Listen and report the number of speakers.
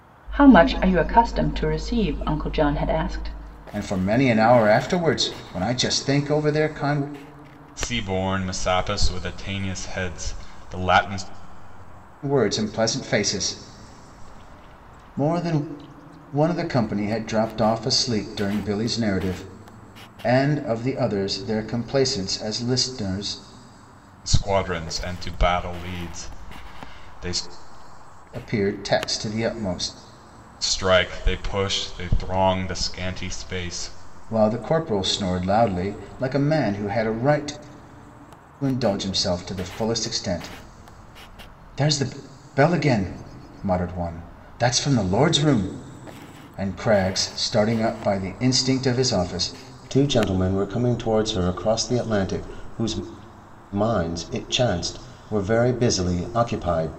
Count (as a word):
three